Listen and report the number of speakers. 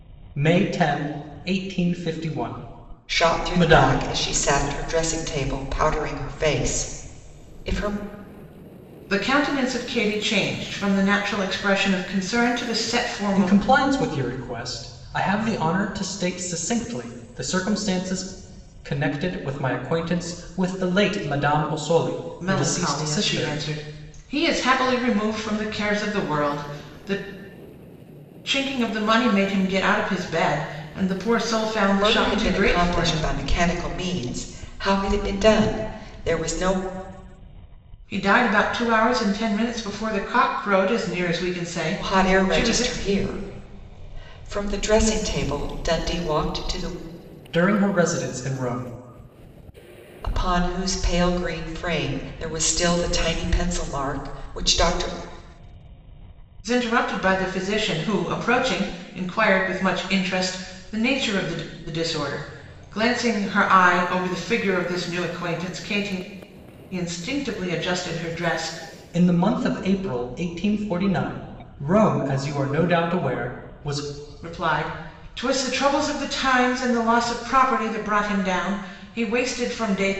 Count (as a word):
three